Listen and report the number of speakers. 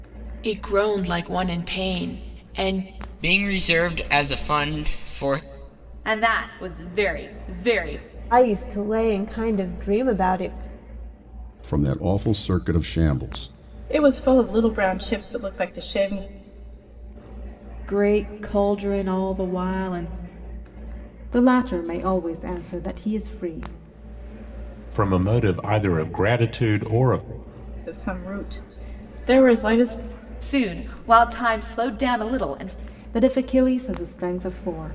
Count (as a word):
nine